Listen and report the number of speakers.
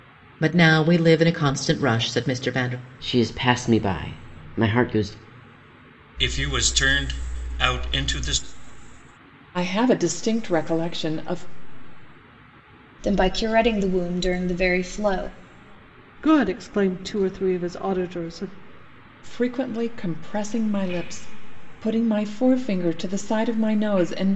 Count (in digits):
6